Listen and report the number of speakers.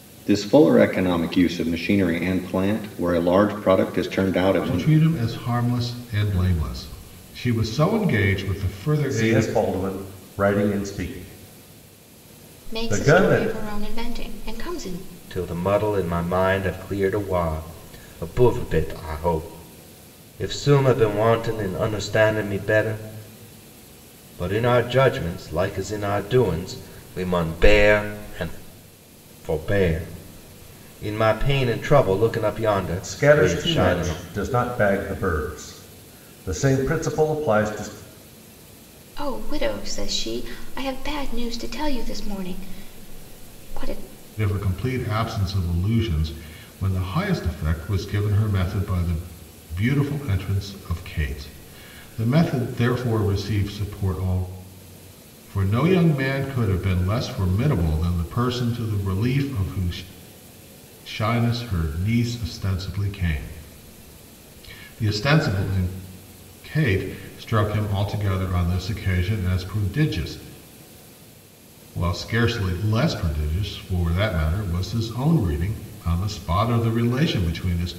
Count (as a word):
five